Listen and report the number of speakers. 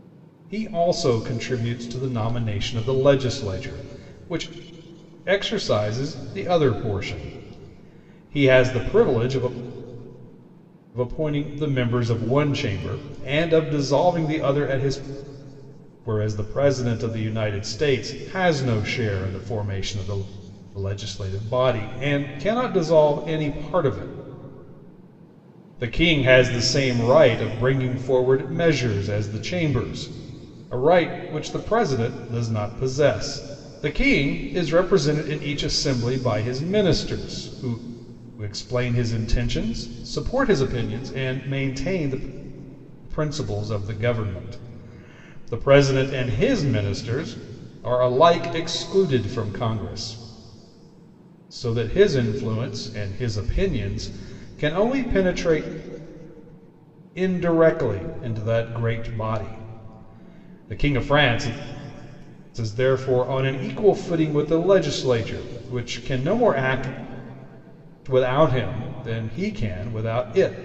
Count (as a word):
one